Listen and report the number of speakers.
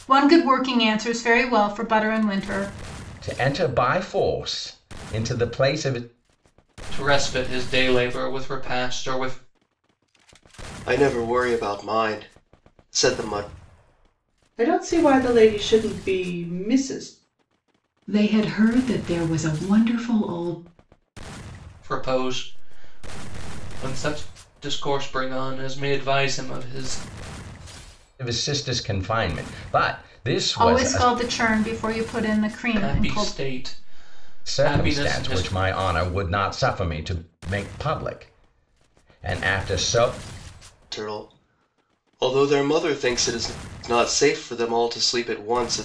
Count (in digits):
6